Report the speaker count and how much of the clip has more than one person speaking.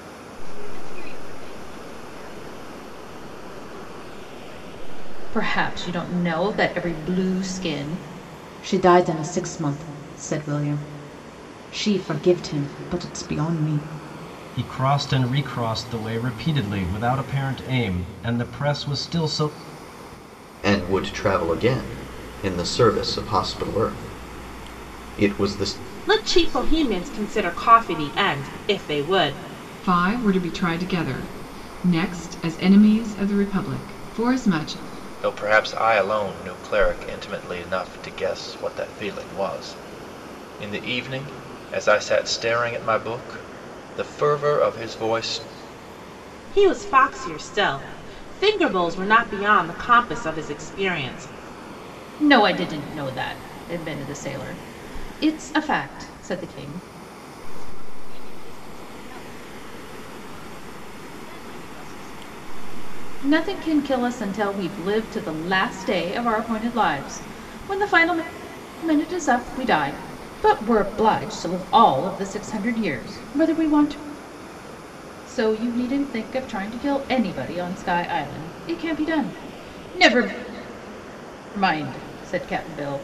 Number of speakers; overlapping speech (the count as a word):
eight, no overlap